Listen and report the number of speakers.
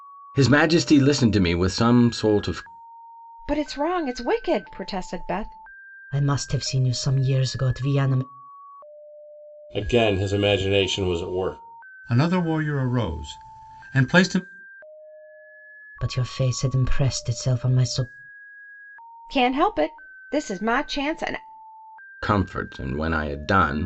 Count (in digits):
5